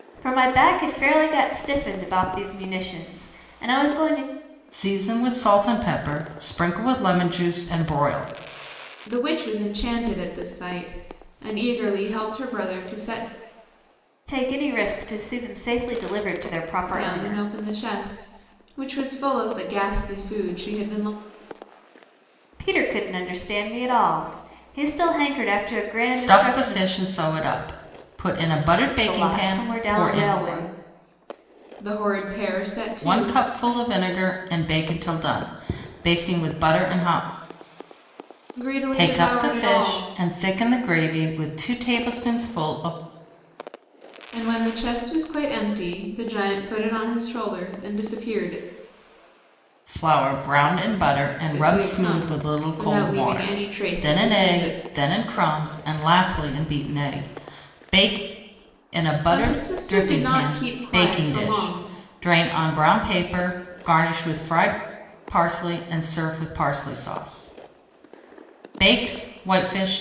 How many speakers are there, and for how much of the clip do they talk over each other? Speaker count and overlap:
3, about 15%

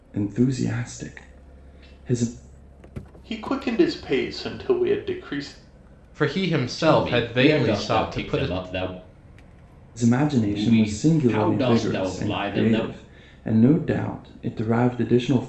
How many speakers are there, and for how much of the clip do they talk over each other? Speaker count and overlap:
4, about 28%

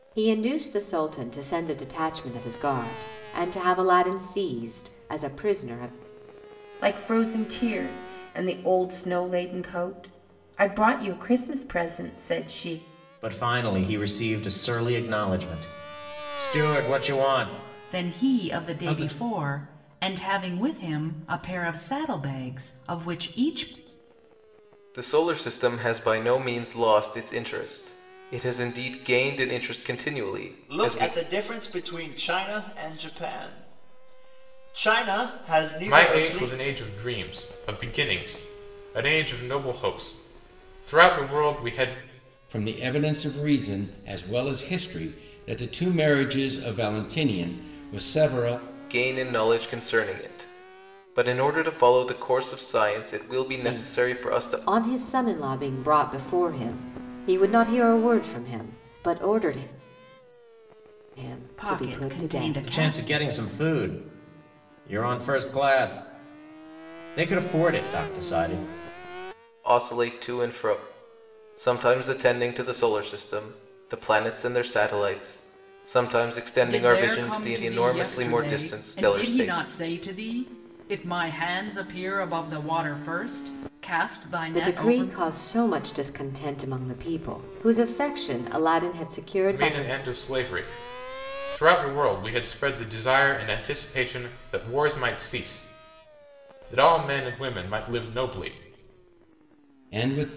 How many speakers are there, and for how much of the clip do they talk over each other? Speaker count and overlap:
8, about 10%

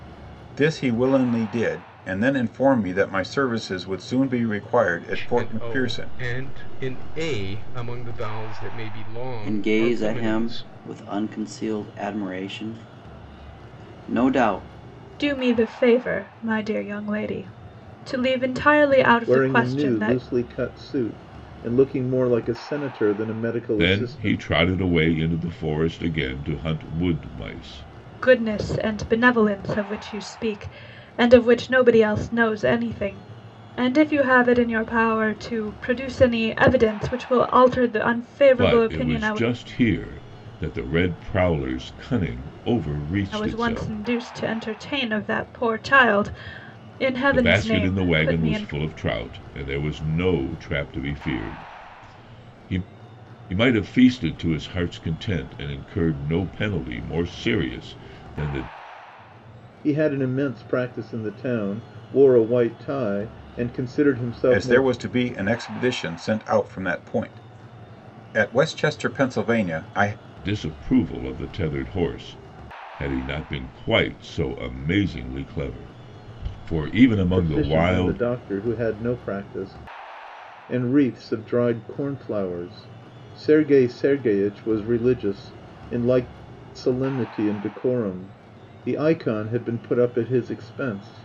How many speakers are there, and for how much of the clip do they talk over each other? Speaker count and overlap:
6, about 10%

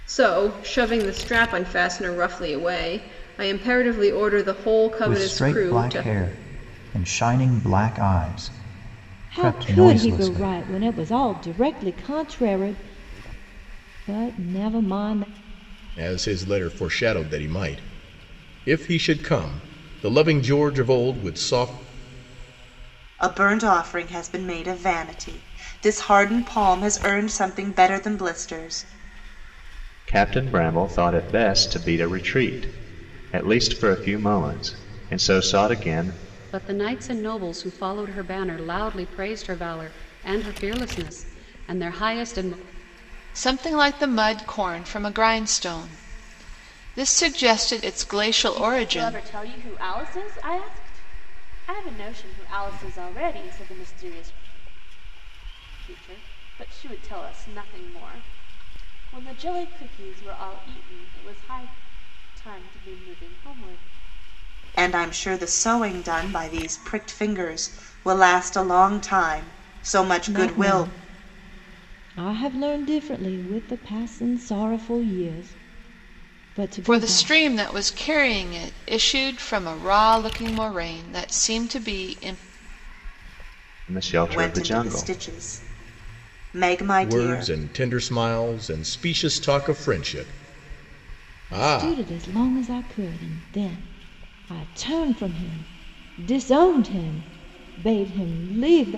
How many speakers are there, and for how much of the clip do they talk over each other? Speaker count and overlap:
9, about 6%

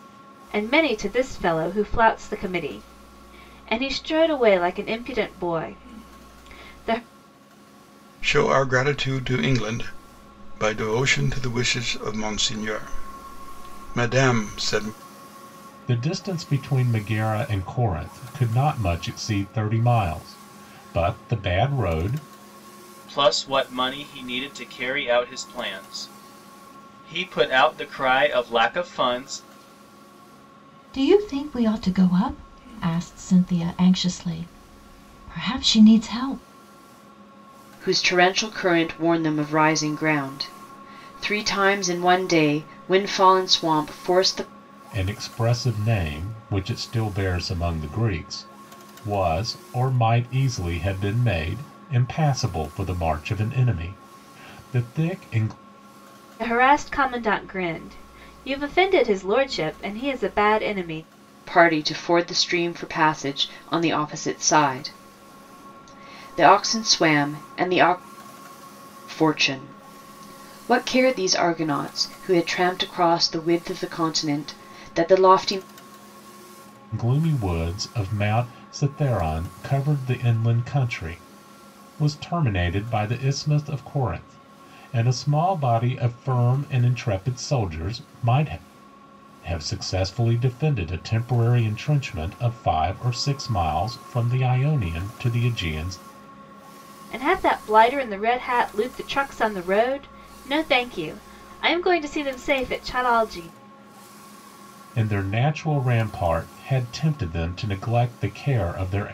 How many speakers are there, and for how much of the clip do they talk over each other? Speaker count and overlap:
6, no overlap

